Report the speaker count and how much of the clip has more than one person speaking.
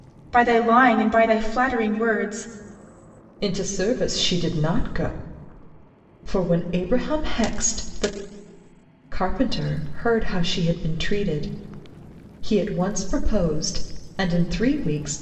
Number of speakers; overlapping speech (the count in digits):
2, no overlap